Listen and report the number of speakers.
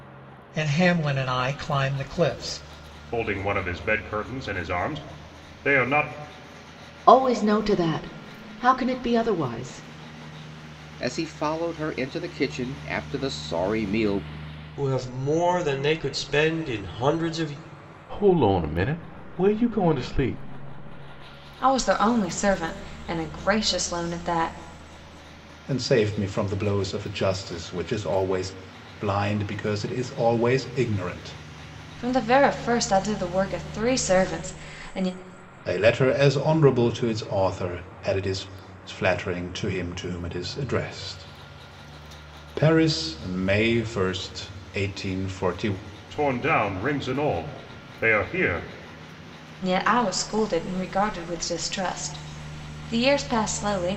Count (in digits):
8